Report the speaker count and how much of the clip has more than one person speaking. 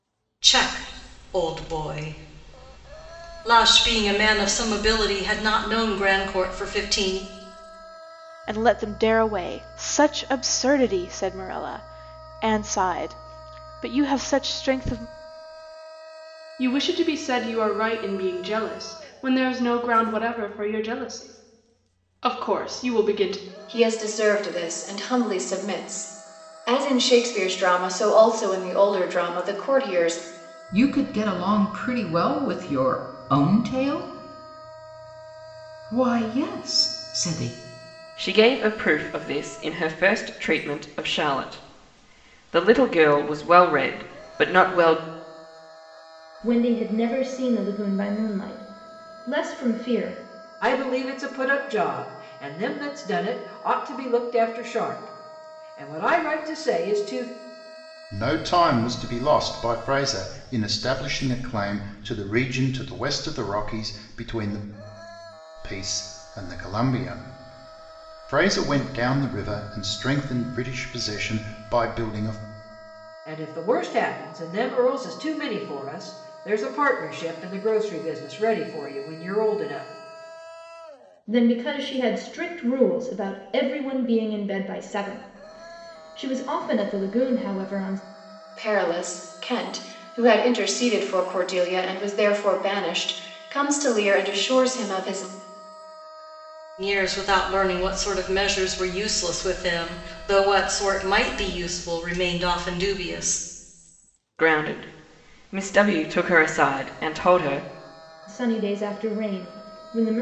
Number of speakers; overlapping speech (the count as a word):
nine, no overlap